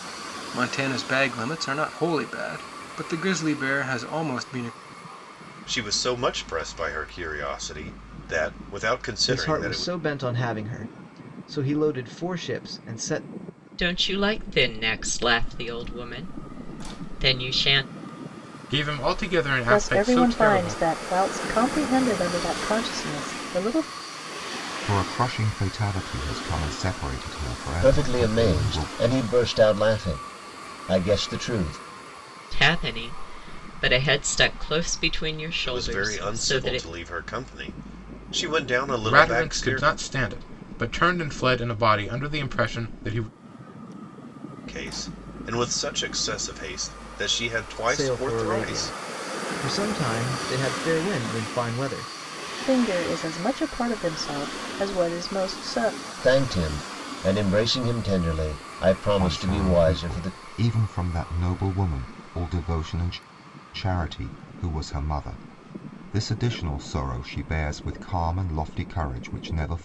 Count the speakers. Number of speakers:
8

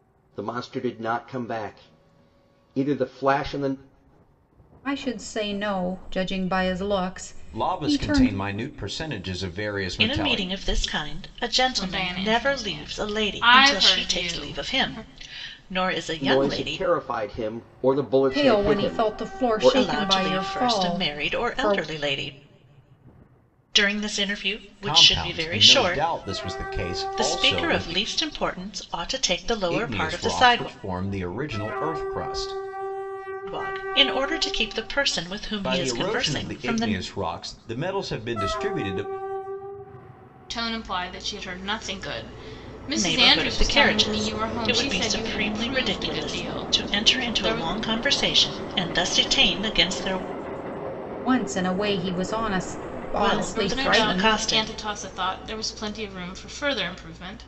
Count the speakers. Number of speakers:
5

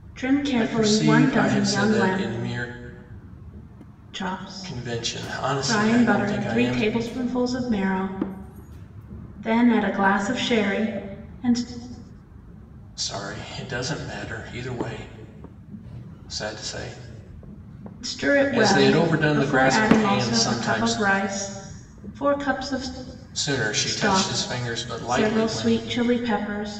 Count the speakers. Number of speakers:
2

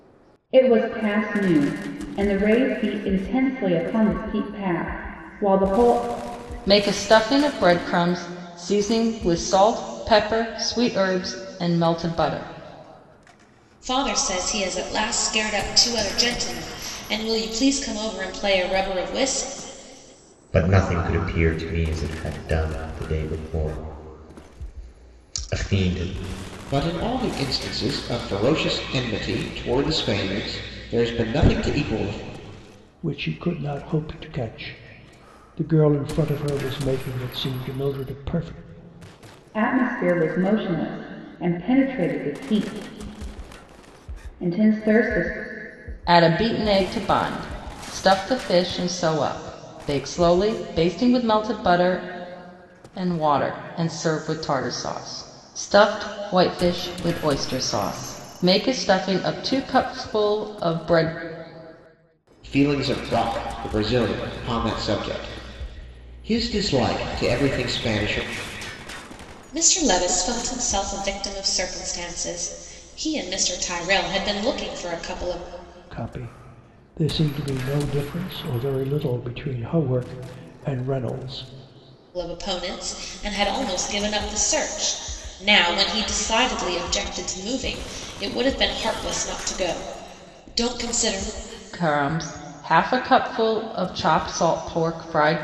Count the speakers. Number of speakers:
6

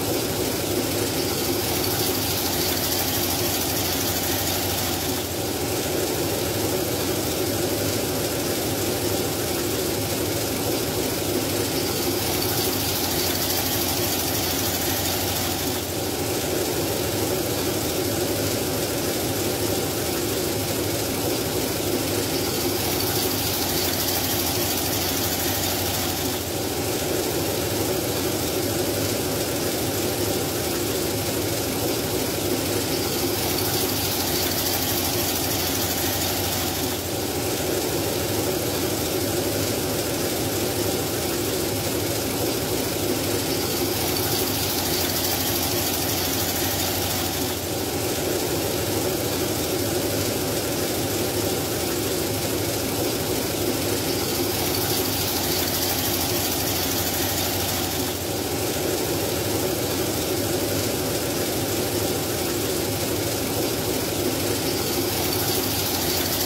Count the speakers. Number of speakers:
0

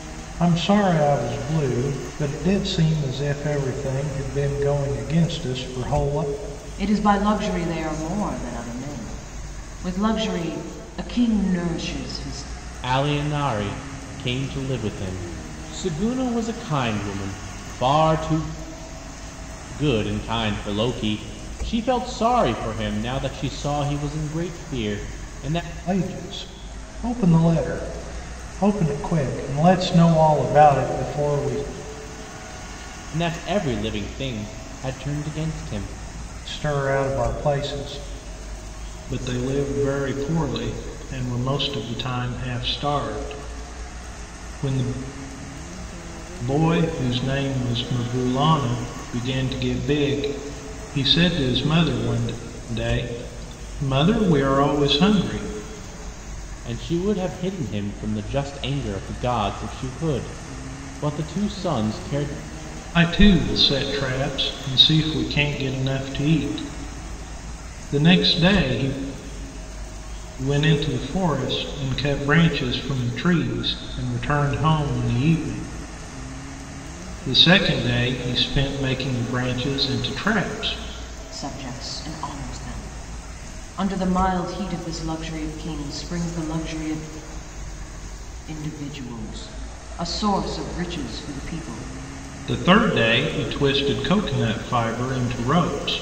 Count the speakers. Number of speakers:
3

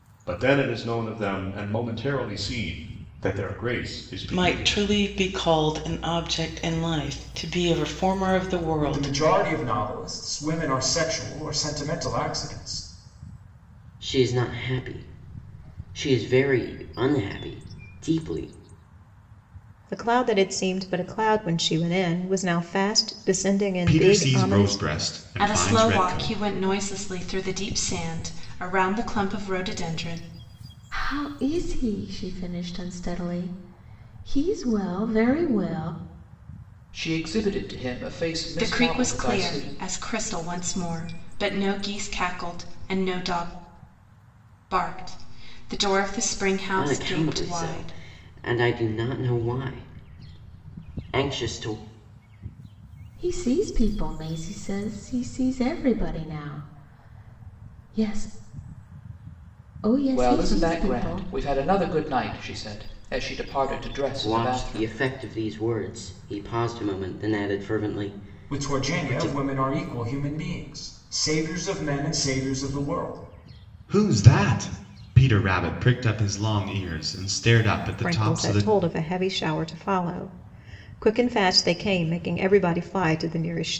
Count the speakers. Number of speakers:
9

